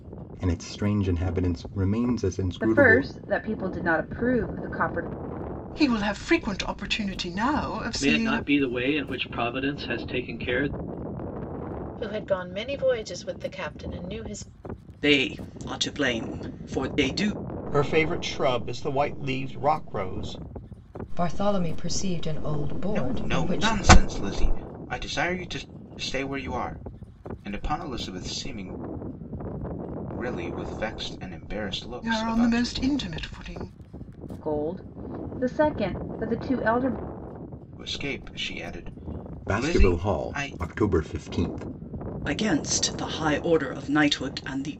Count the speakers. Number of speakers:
9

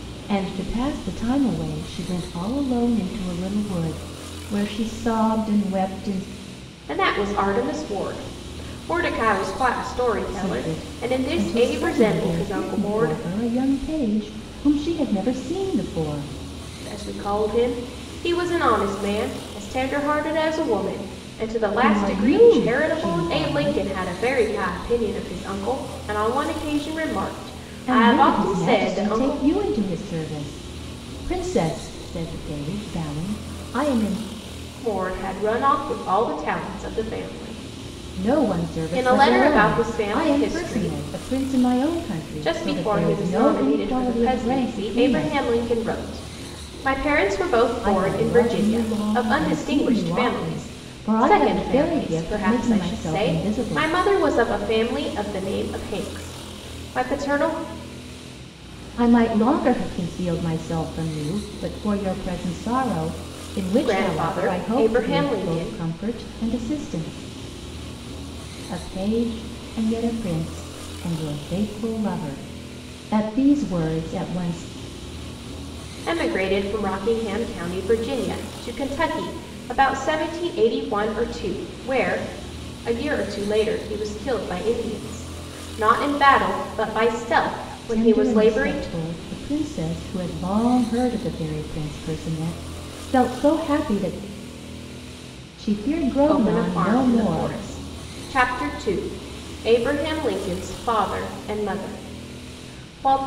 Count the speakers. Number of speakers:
2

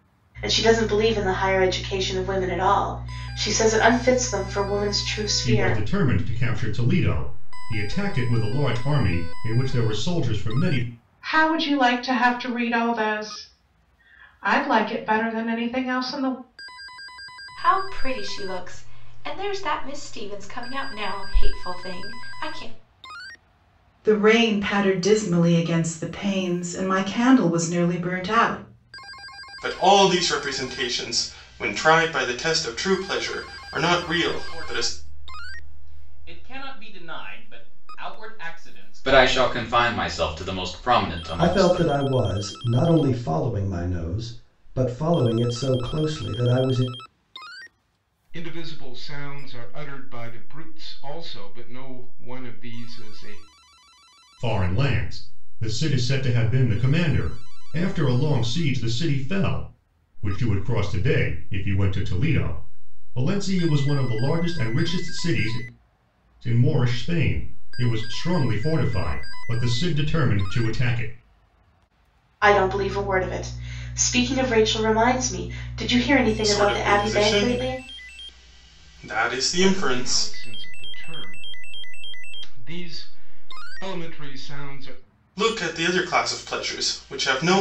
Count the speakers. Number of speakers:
10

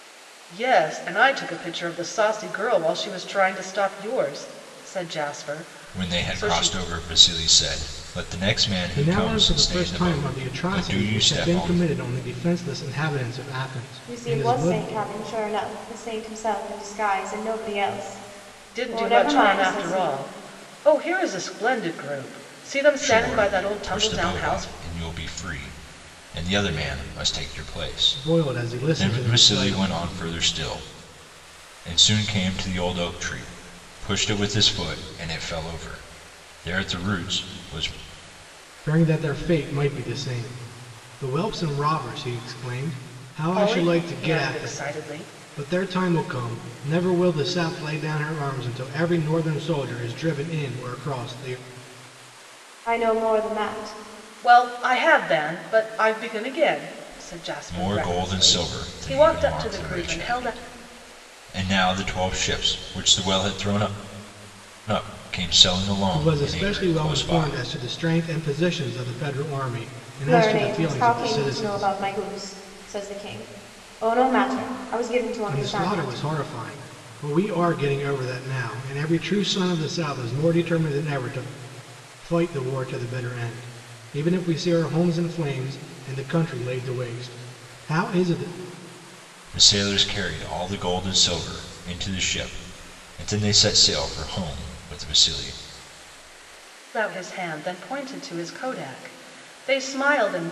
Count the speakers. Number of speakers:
4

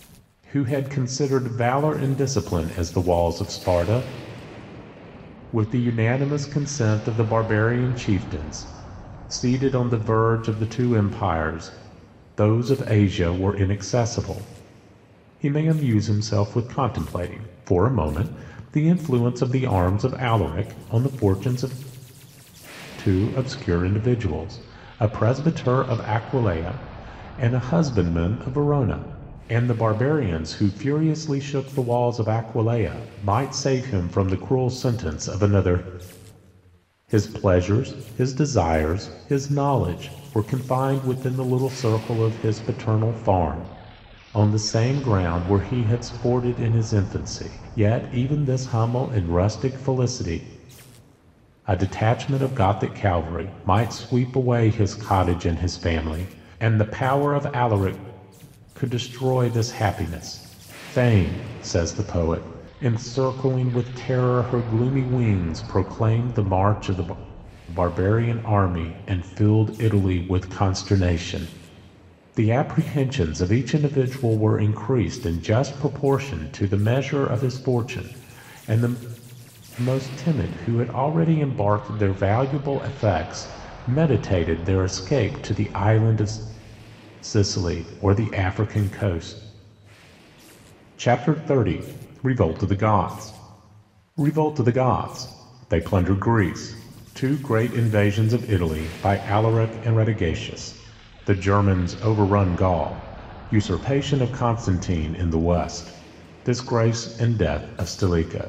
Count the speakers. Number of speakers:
1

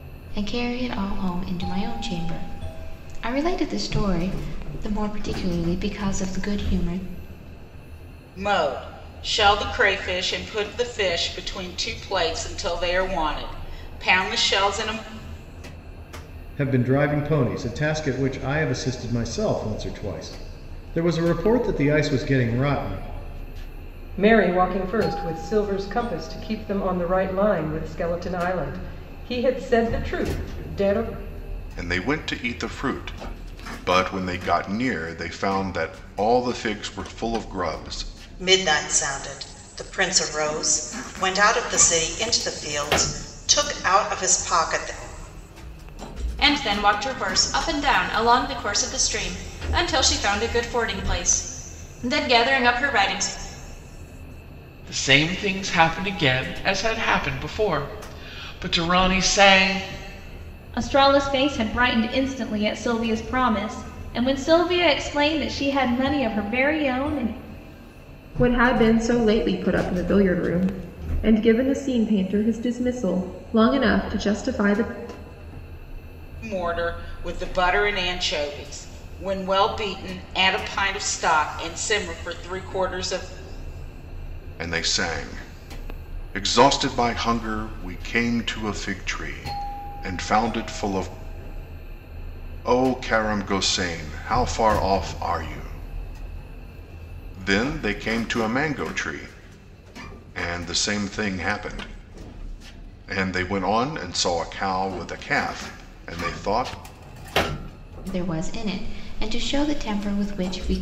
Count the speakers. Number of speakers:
10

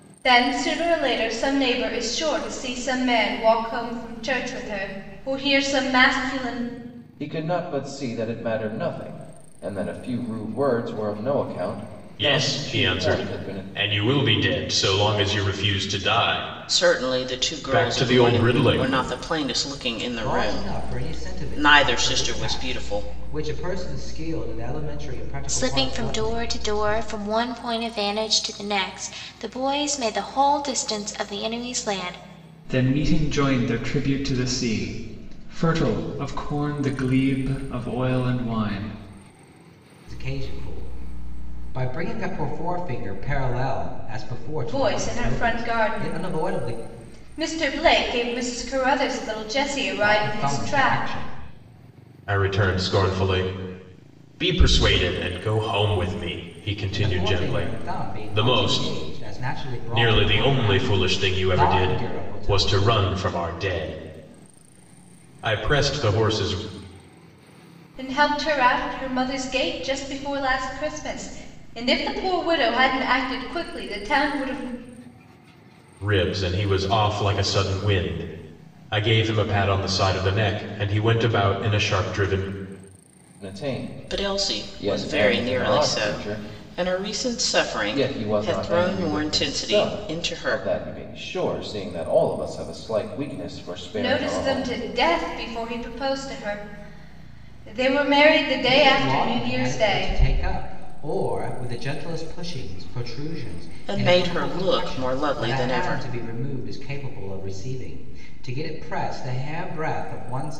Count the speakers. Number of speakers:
7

